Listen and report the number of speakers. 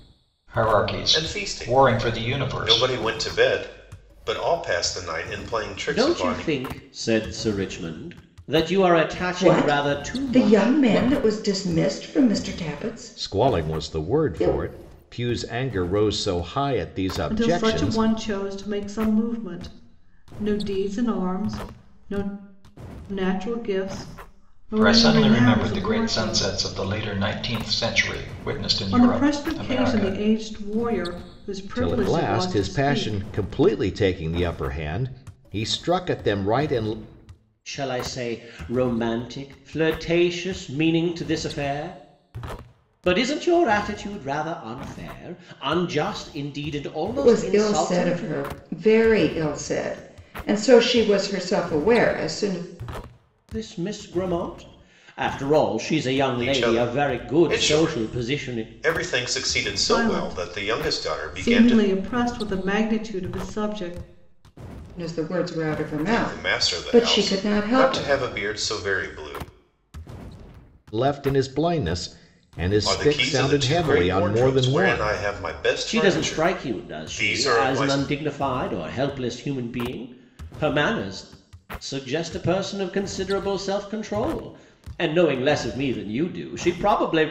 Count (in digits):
6